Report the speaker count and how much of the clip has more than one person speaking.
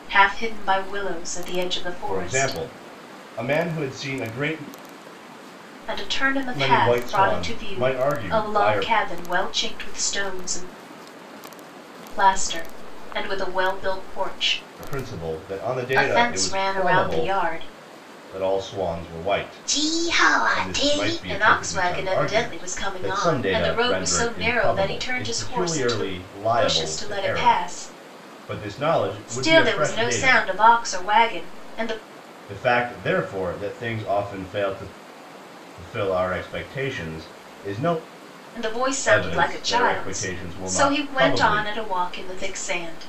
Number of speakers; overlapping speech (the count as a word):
two, about 36%